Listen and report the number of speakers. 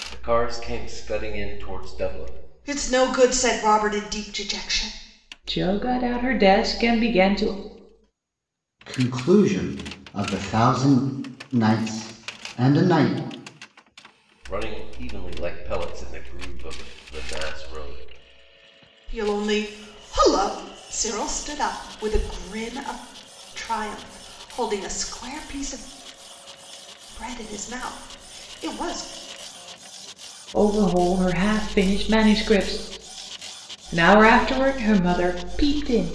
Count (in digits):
4